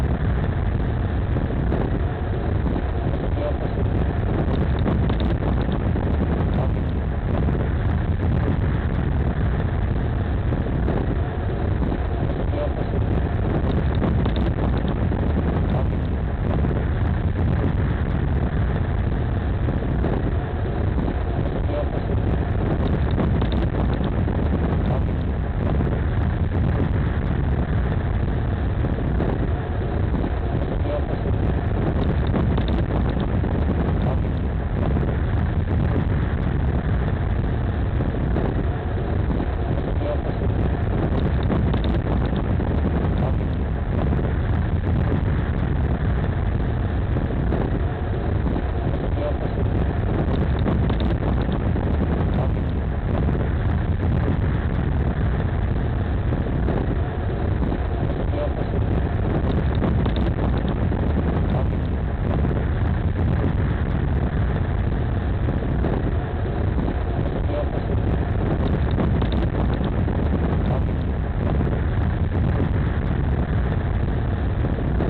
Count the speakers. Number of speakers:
0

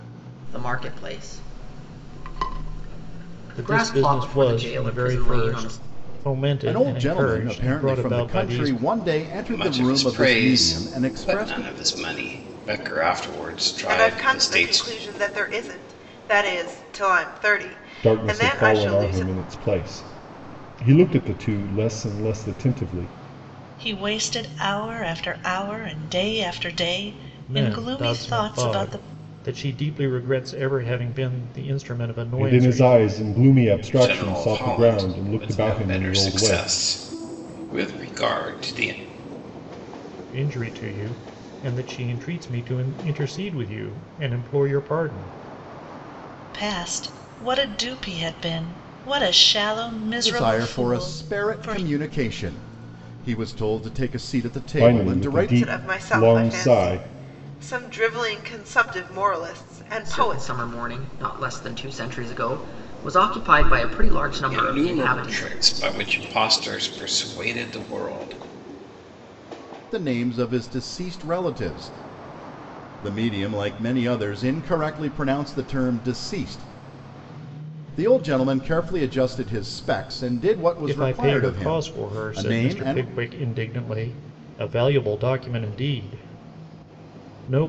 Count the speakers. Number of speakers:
7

